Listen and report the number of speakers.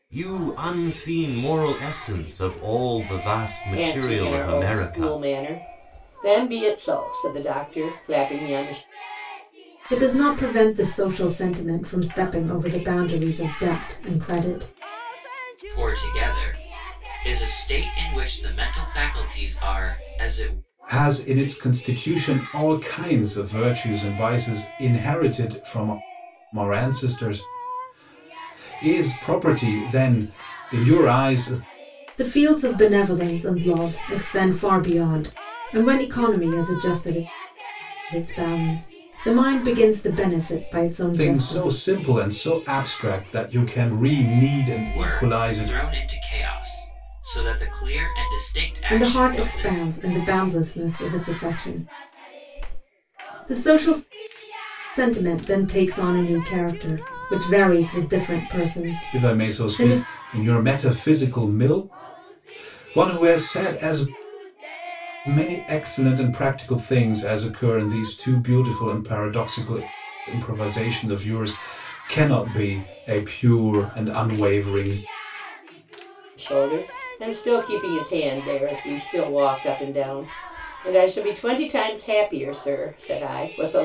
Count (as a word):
five